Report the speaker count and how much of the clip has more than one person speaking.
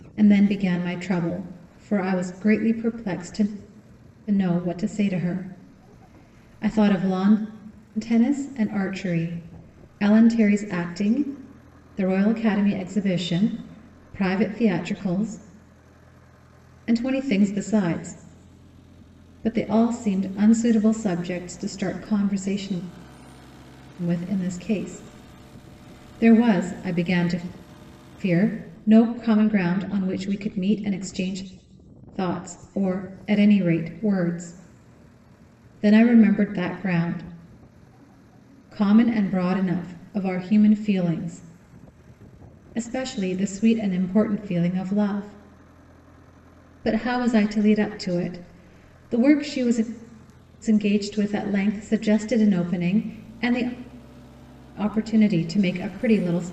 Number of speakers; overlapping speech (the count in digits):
1, no overlap